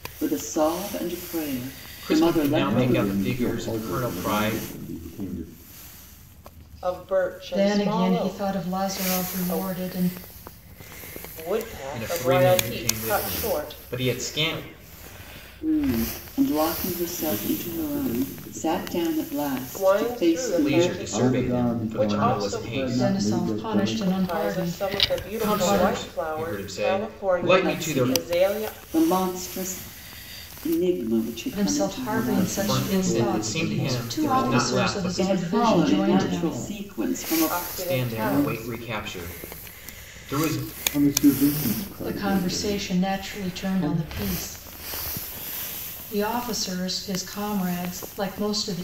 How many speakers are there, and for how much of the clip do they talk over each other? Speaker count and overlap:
five, about 55%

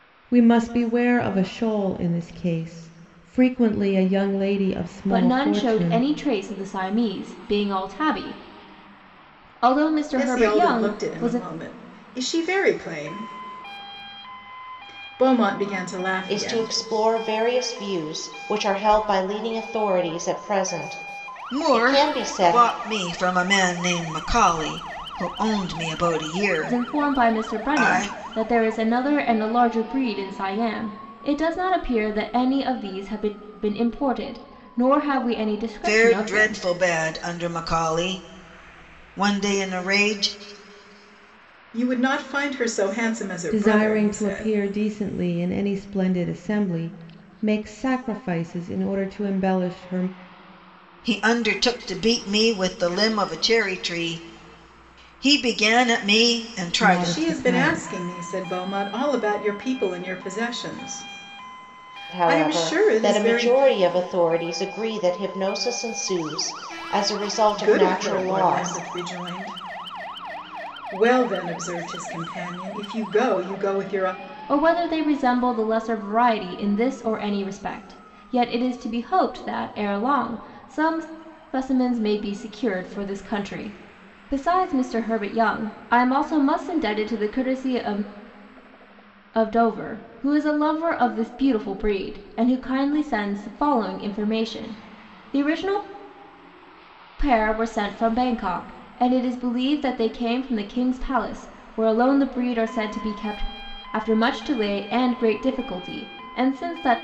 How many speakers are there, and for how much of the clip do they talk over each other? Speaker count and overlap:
five, about 10%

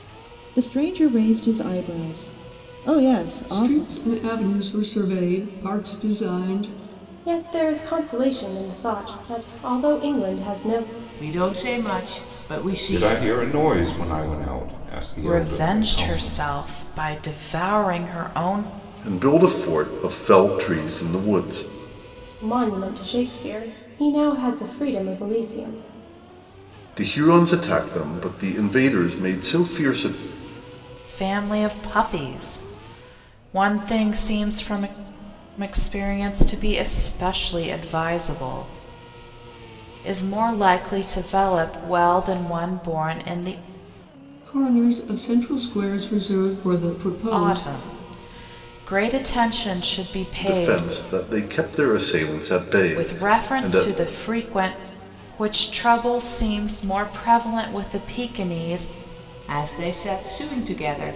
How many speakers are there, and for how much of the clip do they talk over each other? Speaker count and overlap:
seven, about 7%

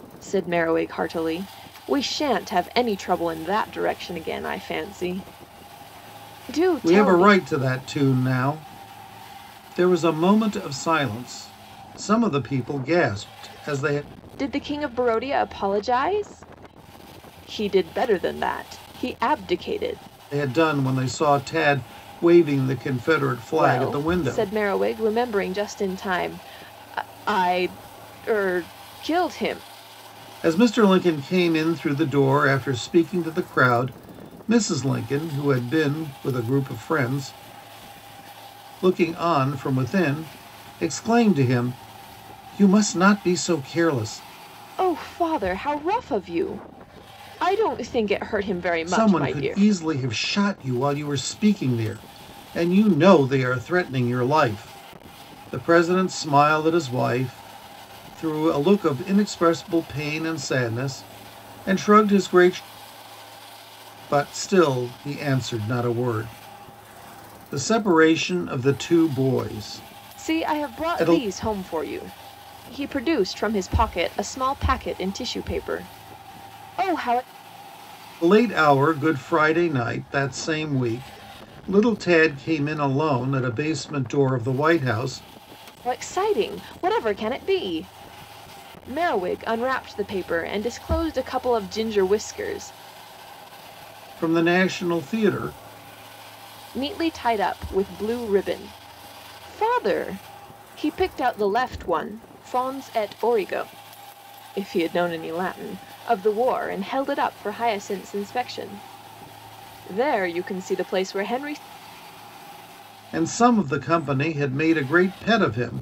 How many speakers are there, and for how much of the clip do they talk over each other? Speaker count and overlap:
two, about 3%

